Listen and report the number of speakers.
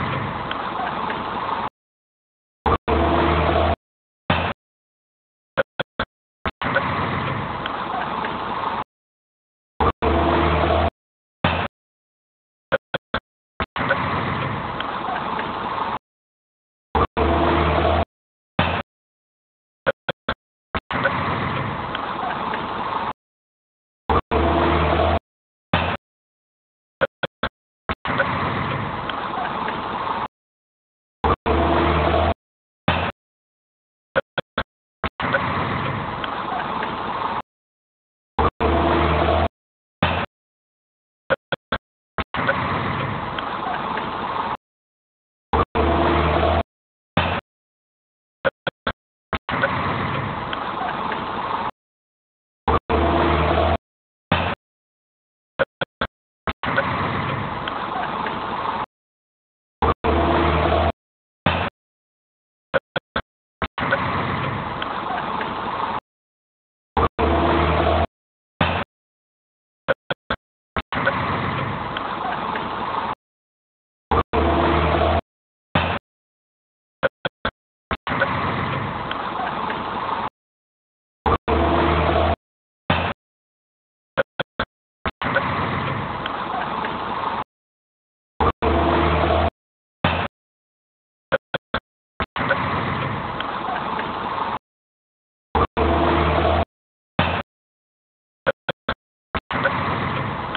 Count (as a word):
zero